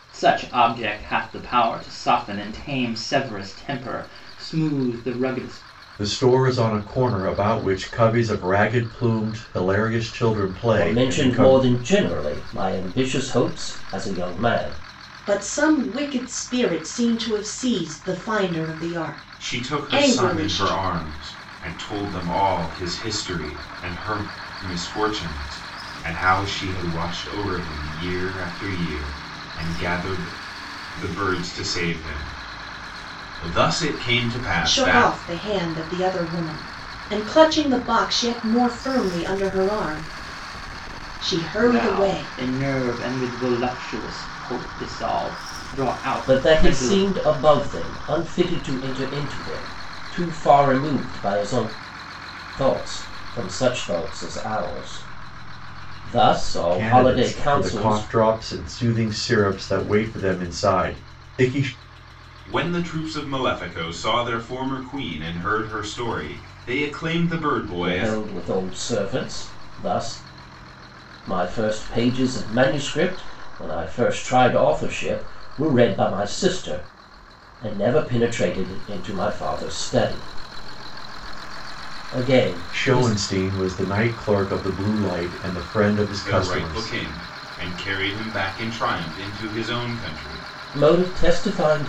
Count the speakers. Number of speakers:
five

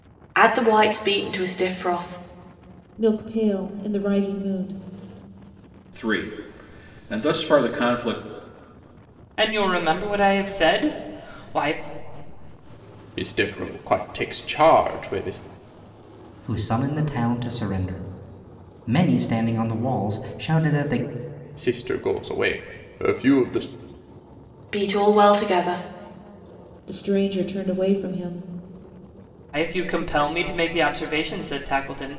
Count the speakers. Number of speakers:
six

